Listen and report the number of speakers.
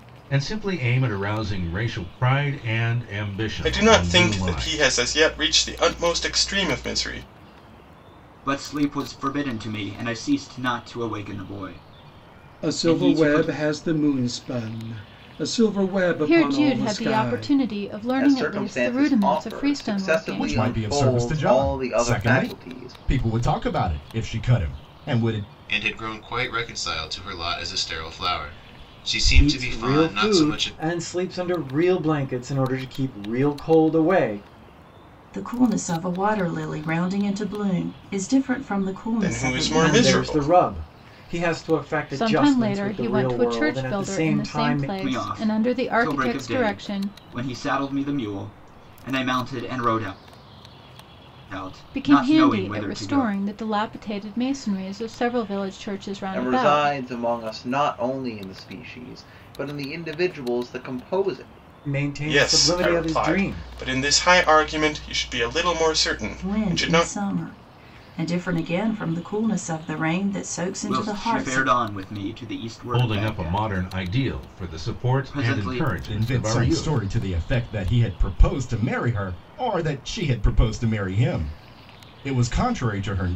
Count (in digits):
10